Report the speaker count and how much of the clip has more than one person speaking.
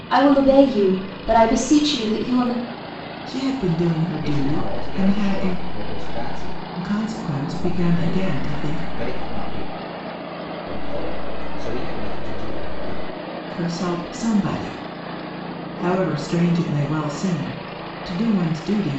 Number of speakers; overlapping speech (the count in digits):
3, about 15%